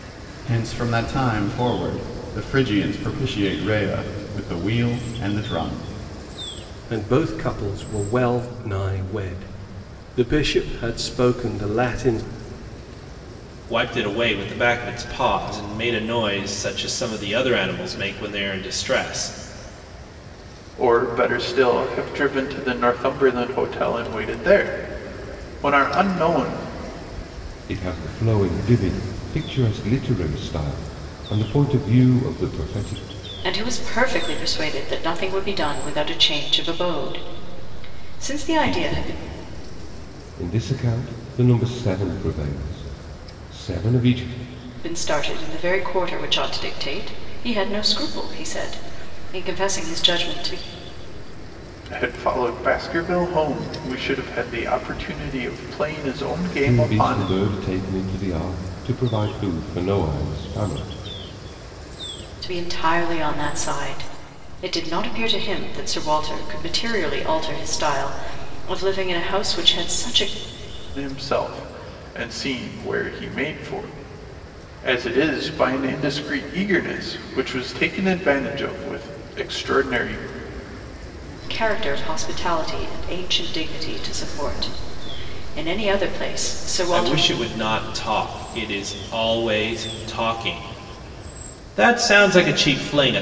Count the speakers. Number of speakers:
six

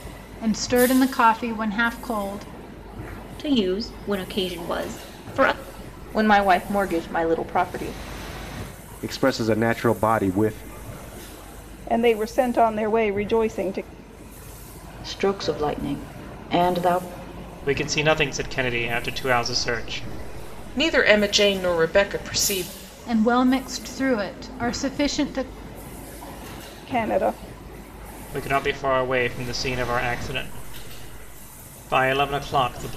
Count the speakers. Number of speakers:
eight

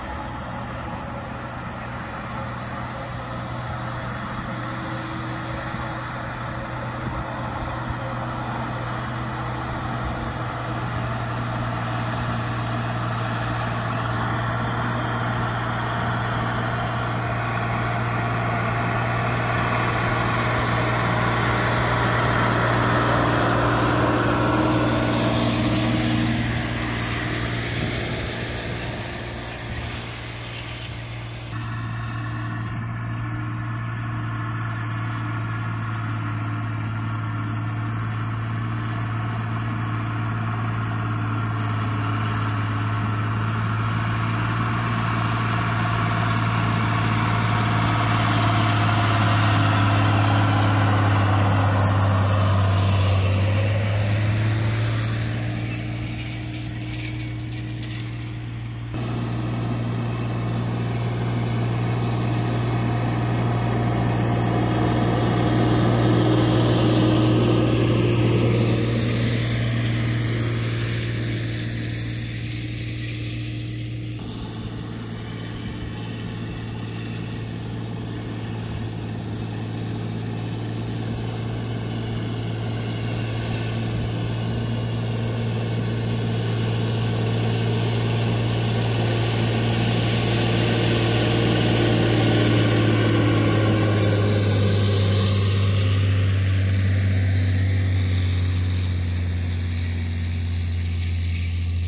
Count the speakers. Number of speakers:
zero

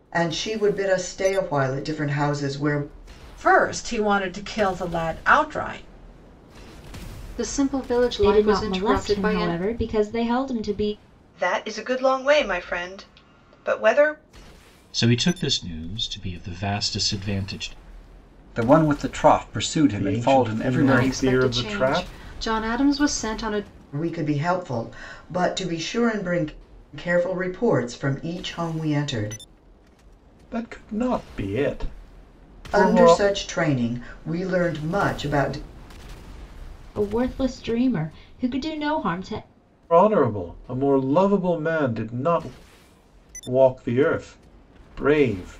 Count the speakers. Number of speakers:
eight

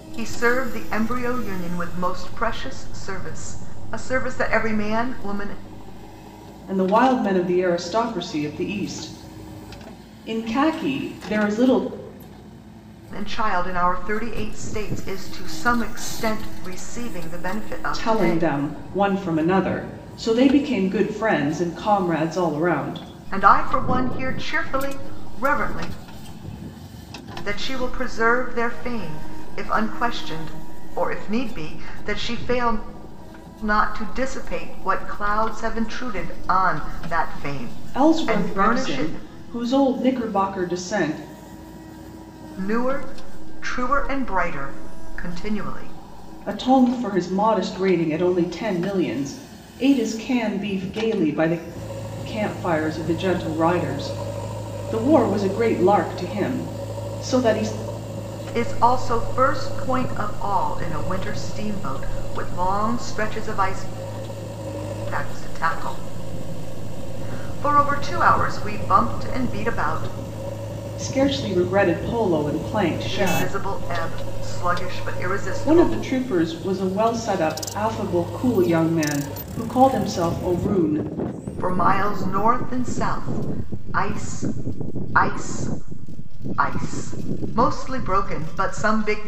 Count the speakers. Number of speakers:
two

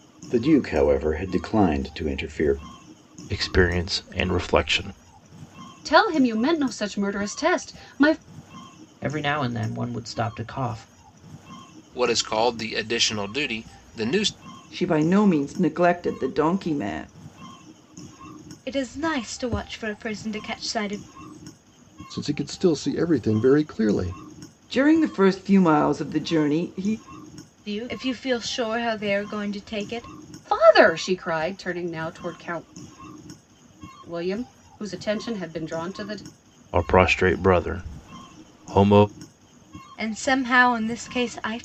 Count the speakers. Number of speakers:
eight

